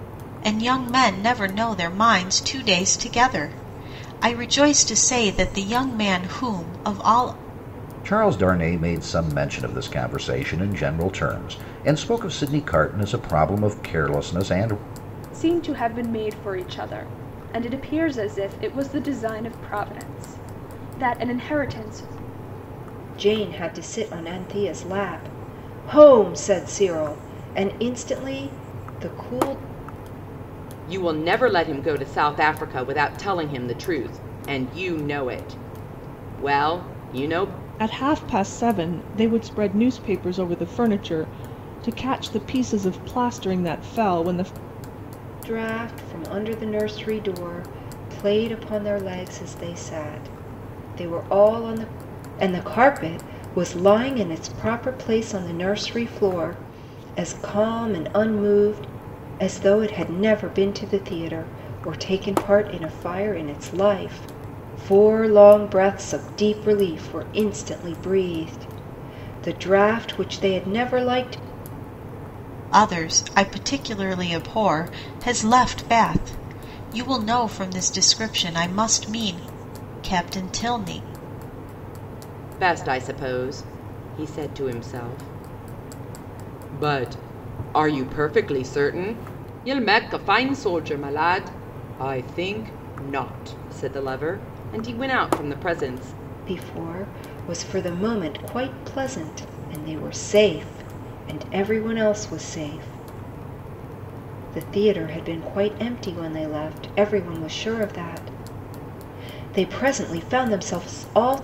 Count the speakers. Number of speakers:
6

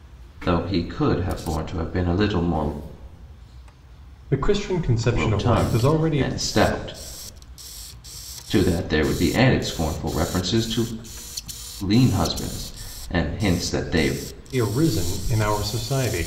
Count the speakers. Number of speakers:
2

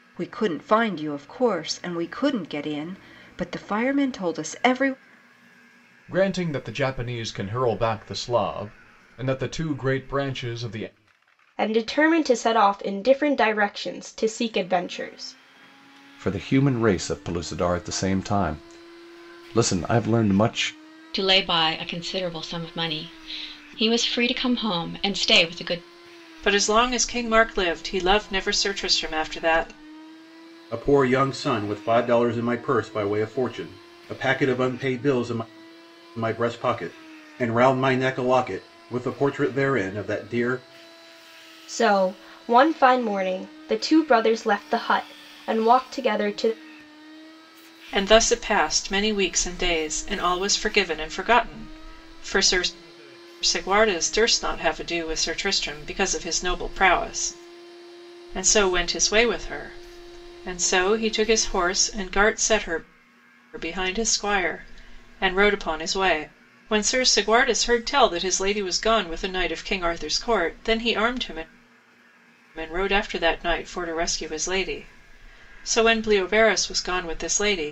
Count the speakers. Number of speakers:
7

